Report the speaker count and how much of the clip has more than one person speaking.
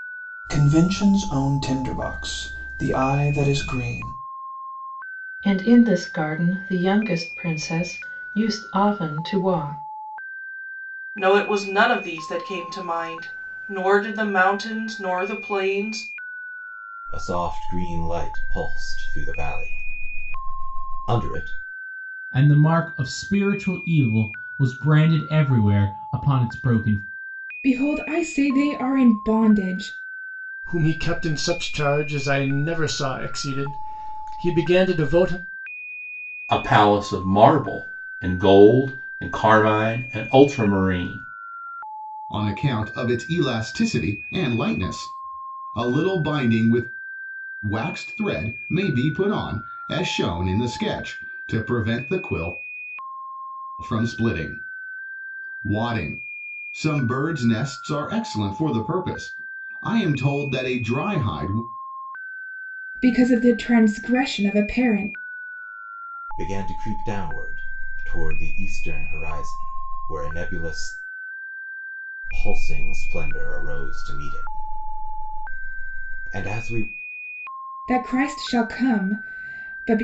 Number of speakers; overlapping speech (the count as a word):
nine, no overlap